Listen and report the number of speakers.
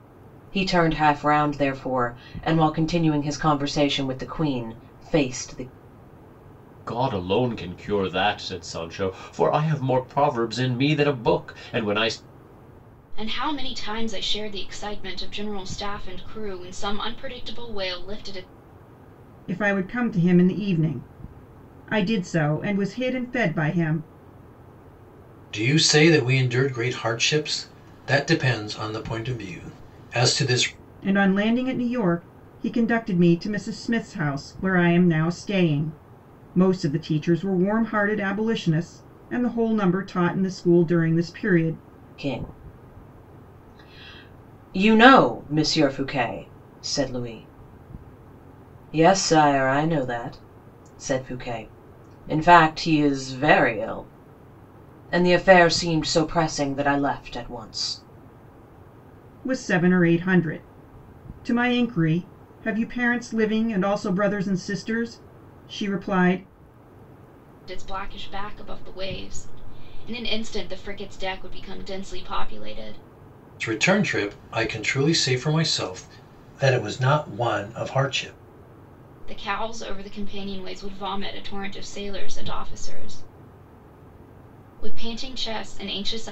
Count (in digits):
5